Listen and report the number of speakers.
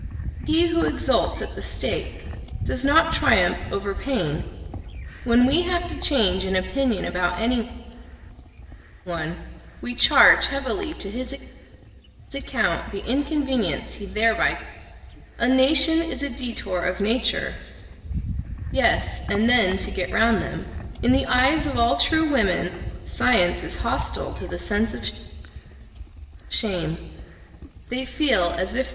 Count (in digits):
1